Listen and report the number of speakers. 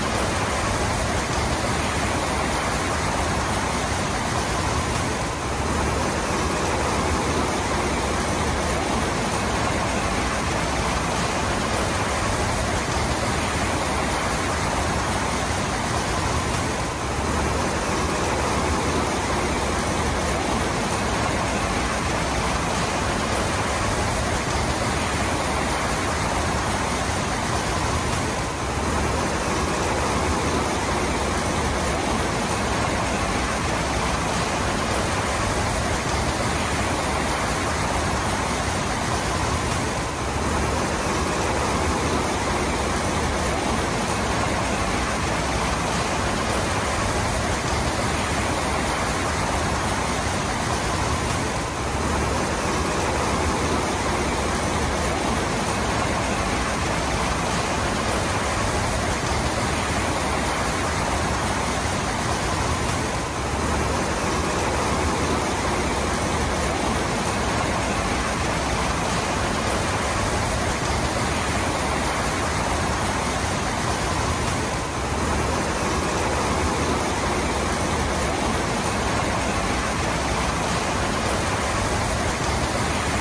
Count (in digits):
0